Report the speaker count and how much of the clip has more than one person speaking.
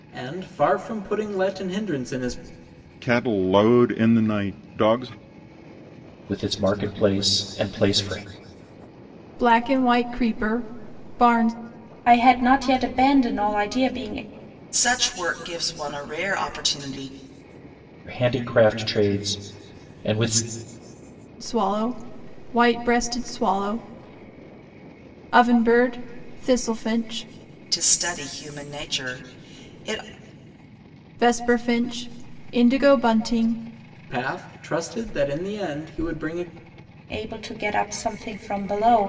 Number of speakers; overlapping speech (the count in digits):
6, no overlap